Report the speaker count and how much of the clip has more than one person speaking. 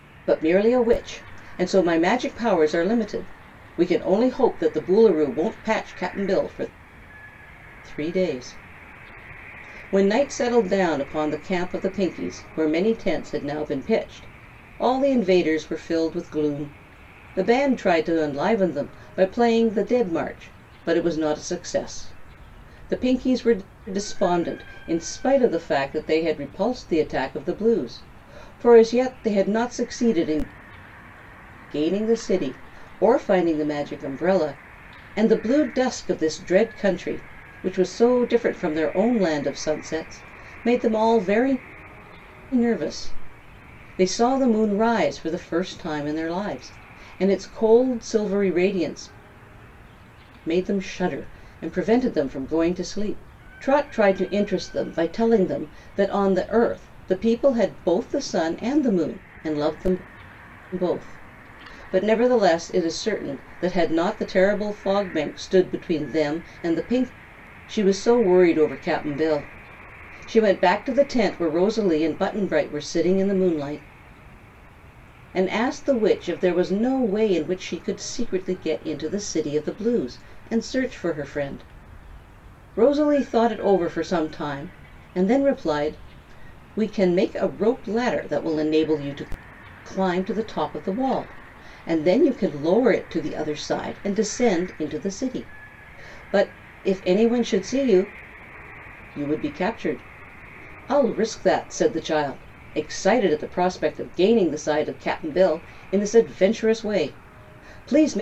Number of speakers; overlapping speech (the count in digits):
1, no overlap